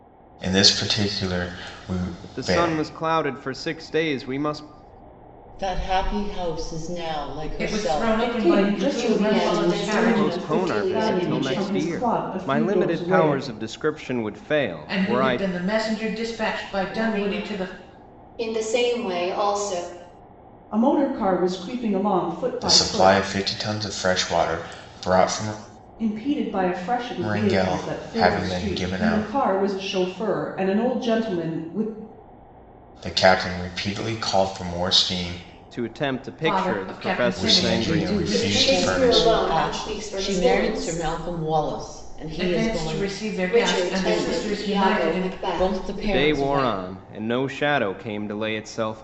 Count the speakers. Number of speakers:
six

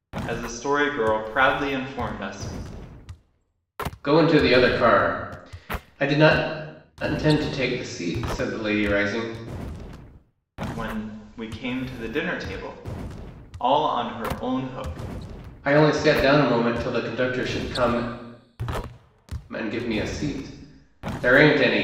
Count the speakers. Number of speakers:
two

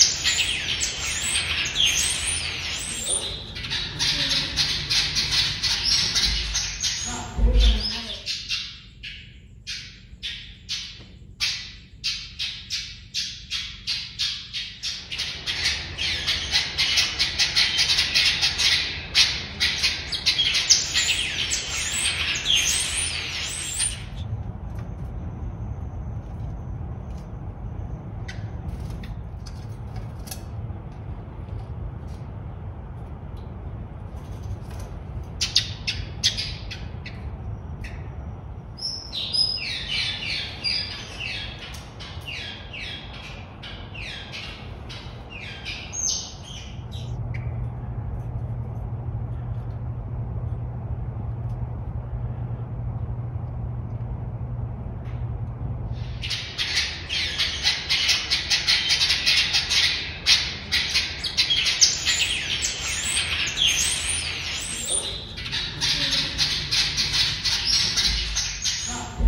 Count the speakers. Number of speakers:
zero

